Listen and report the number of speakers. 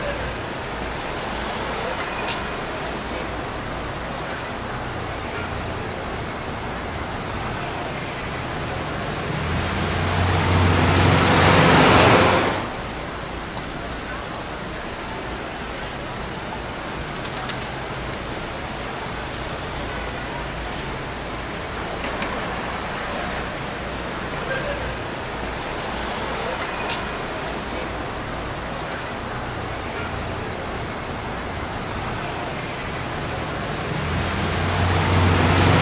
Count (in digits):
0